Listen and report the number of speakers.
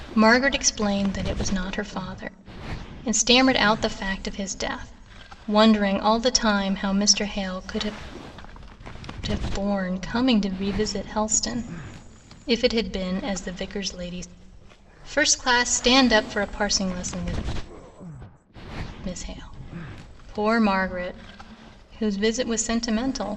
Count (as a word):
one